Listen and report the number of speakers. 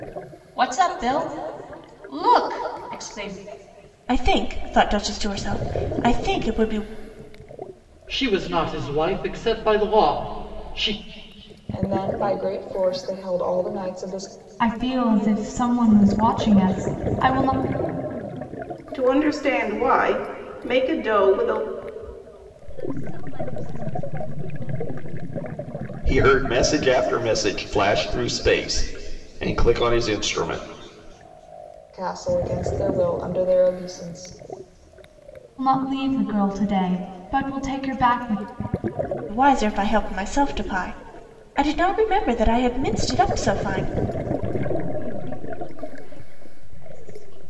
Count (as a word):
eight